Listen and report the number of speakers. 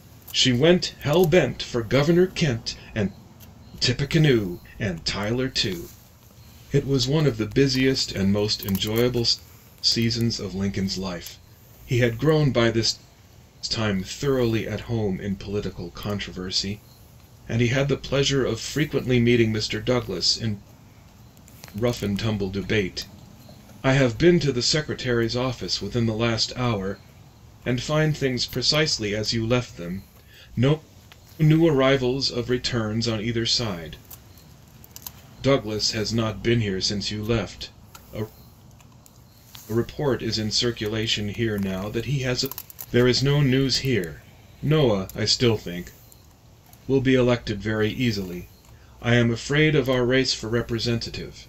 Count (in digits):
1